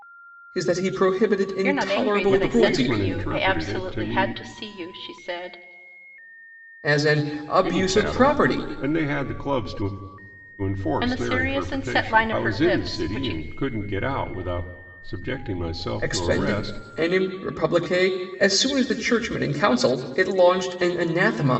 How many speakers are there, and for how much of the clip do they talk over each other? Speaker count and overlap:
3, about 33%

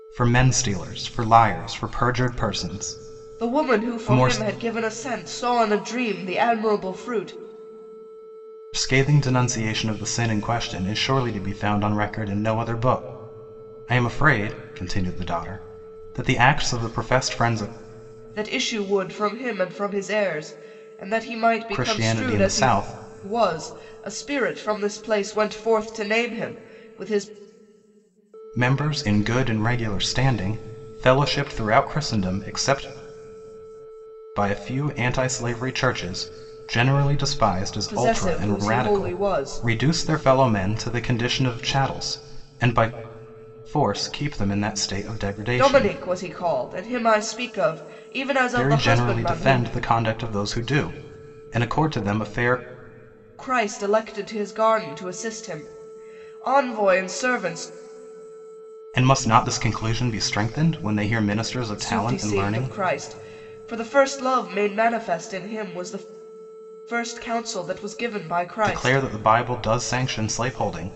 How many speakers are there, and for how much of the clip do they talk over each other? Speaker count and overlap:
2, about 10%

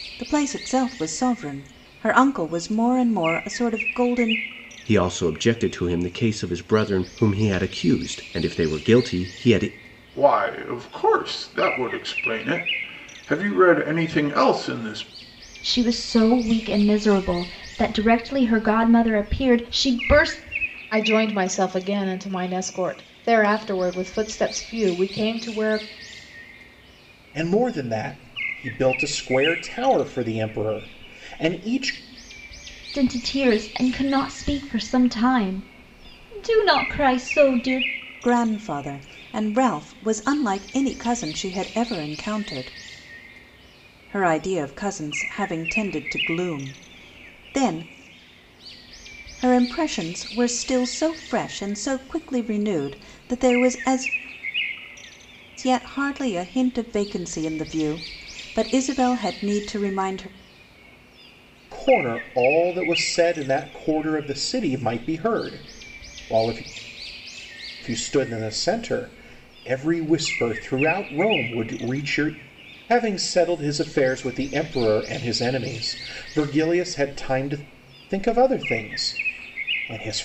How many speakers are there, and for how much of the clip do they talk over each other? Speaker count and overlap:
6, no overlap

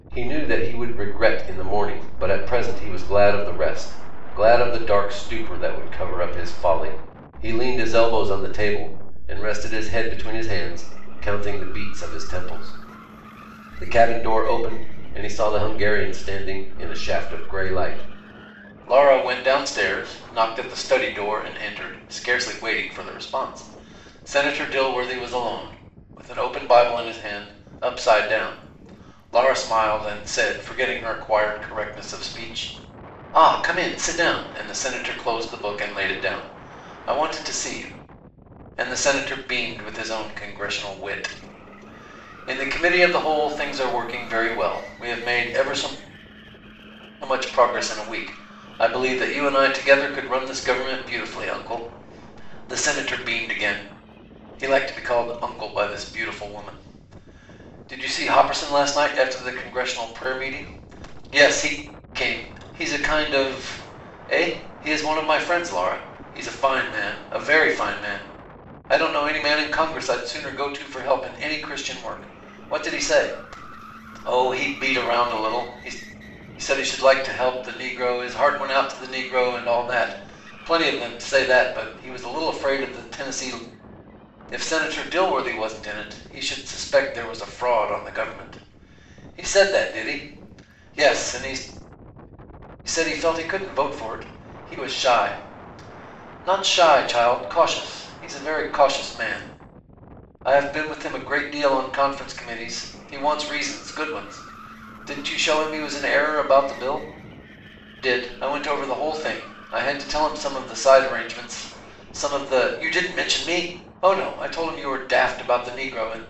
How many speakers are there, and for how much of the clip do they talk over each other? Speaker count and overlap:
1, no overlap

